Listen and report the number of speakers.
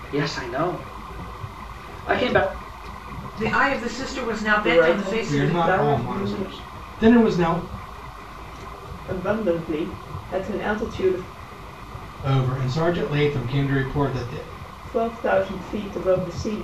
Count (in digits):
4